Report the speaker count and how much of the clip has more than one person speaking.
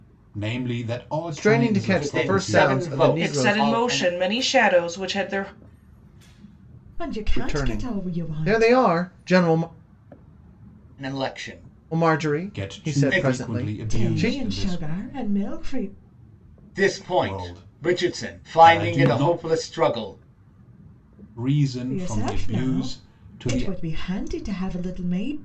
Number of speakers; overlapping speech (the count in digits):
5, about 44%